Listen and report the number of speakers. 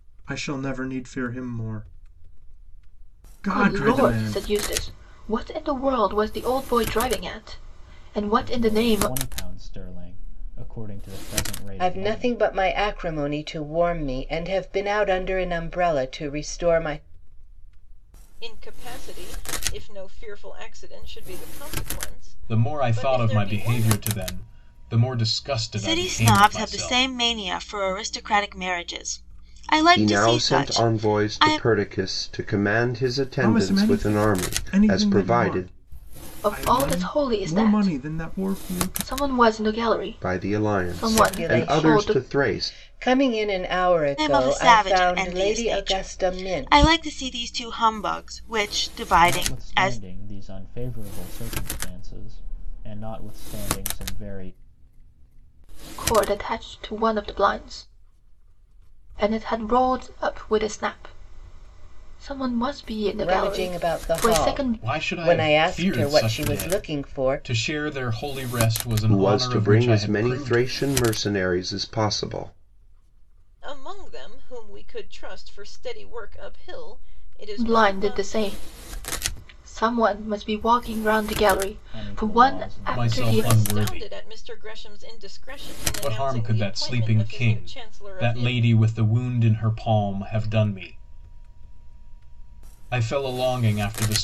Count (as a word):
eight